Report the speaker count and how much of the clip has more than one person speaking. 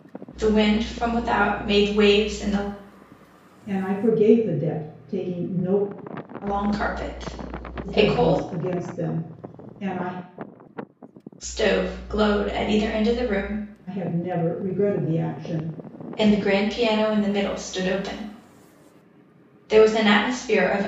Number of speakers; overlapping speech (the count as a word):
two, about 3%